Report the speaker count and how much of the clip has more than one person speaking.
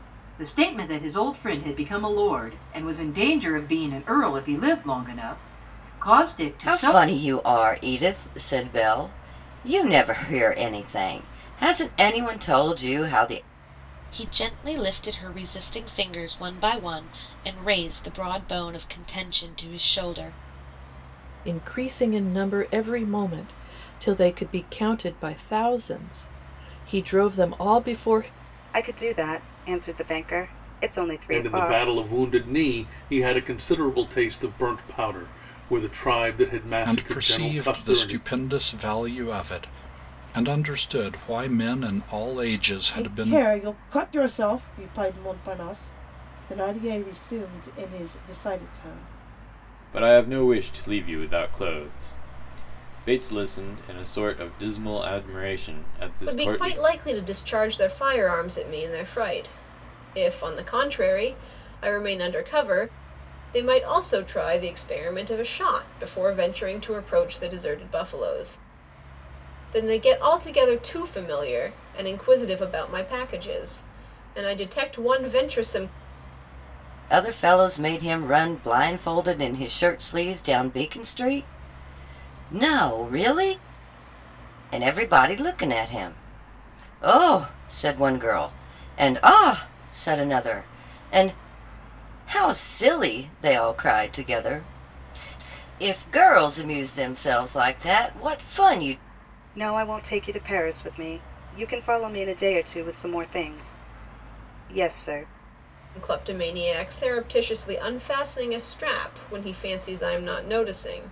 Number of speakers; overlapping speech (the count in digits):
10, about 3%